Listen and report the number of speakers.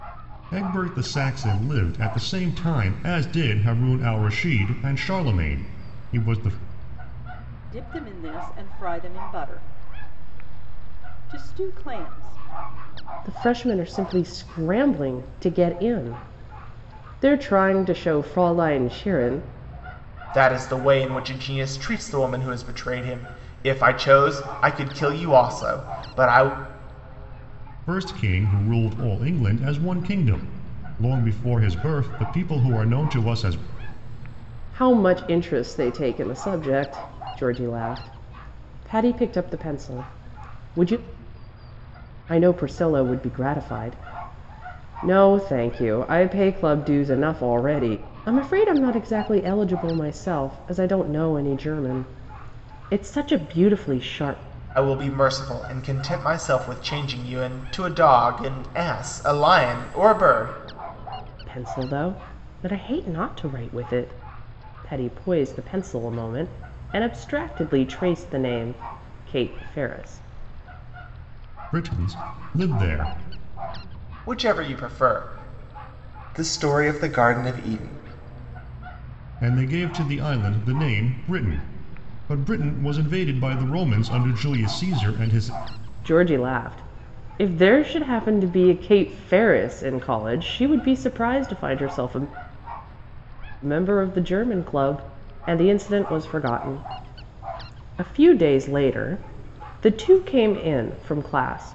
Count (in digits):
4